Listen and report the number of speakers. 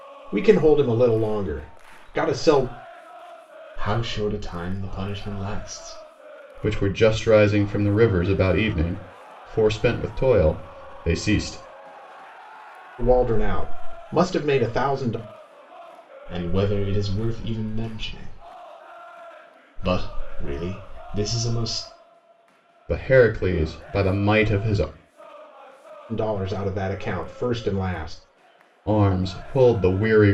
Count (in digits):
3